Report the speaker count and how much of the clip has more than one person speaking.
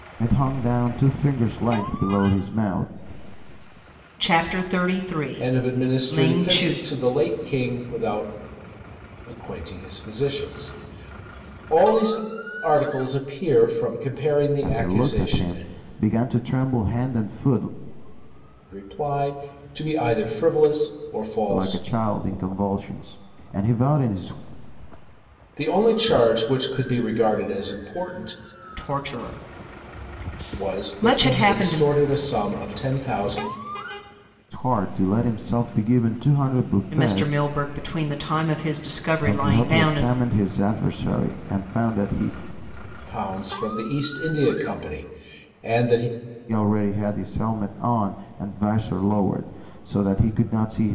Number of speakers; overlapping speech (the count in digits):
3, about 11%